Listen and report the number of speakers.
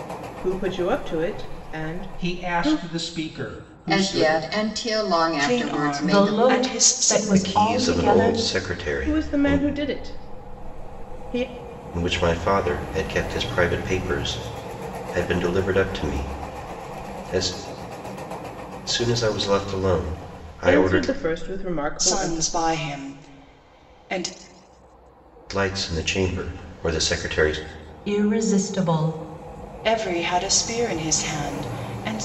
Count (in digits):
6